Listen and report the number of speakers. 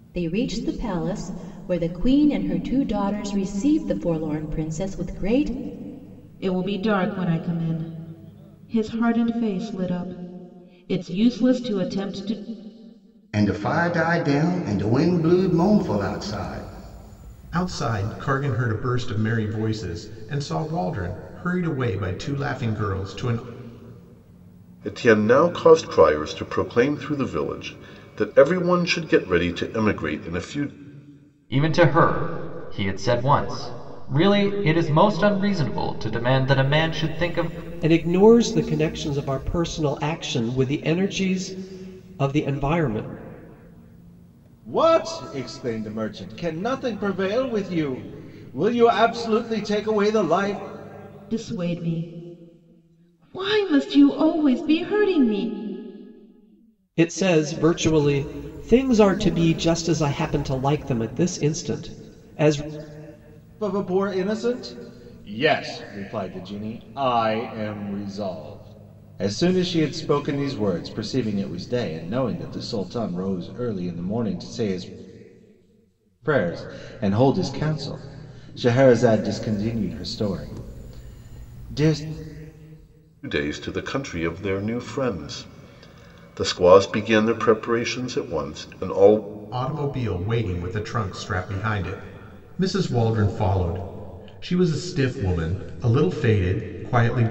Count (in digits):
8